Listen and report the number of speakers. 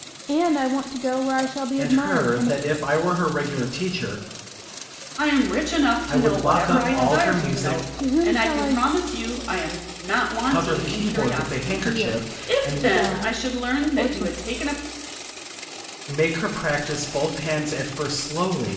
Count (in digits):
3